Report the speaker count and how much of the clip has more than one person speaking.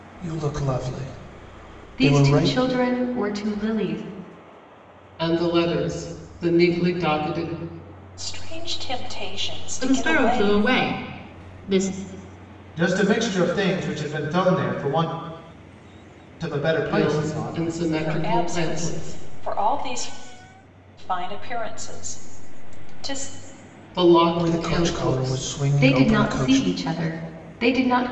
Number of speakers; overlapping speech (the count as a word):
six, about 20%